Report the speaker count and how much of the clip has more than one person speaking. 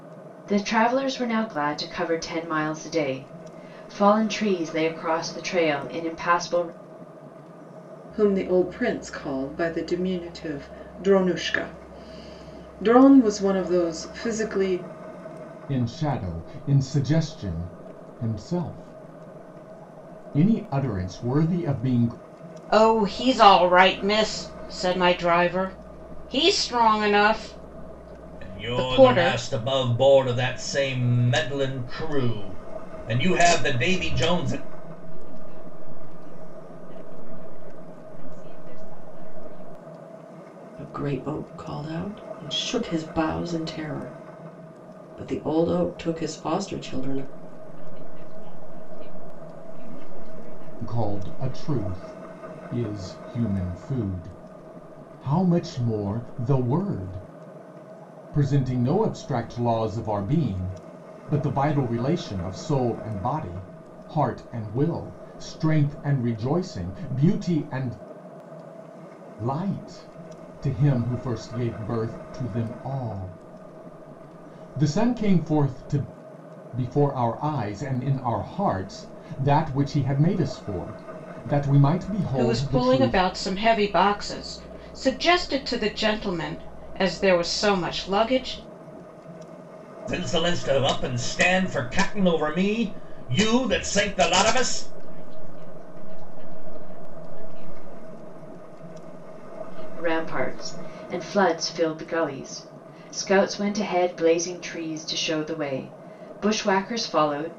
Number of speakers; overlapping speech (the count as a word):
seven, about 6%